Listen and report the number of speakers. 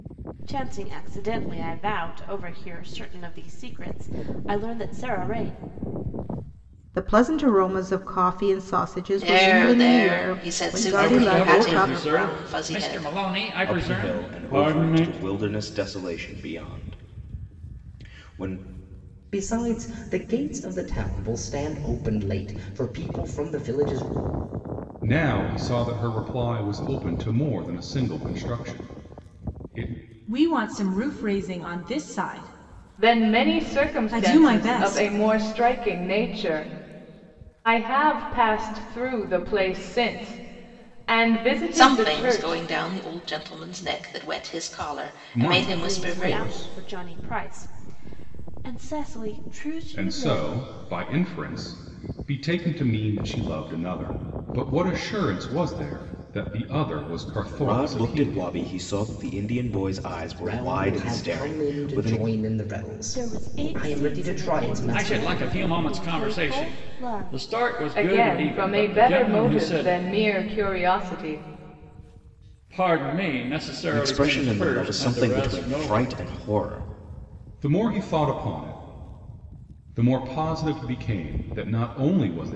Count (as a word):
nine